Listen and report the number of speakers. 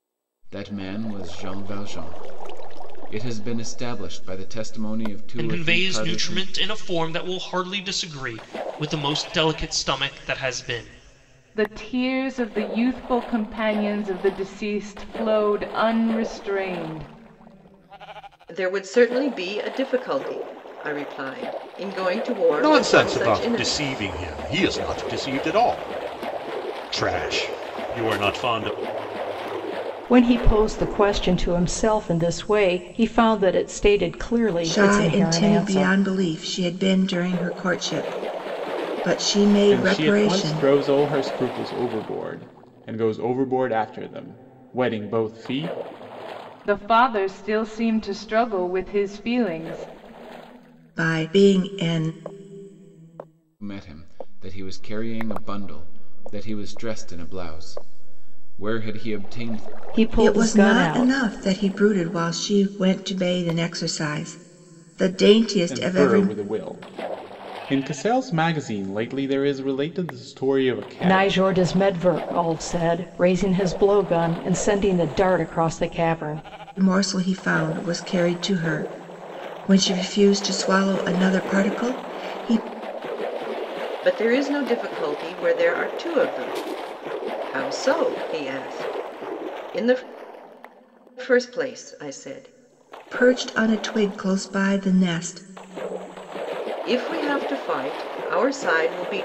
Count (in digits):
8